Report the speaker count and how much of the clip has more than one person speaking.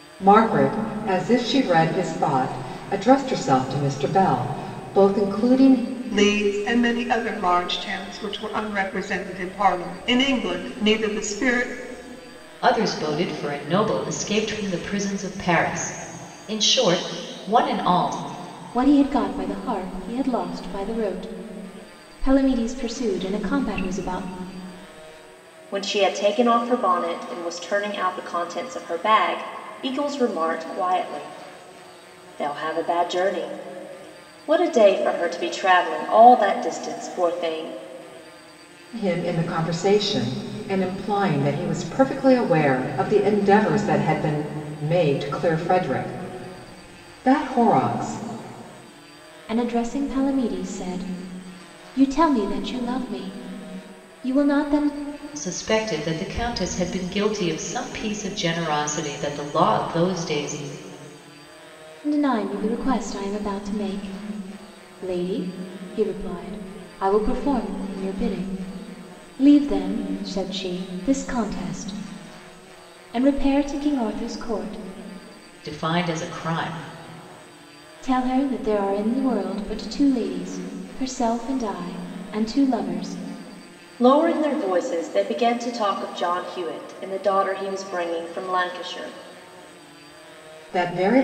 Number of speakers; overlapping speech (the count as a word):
five, no overlap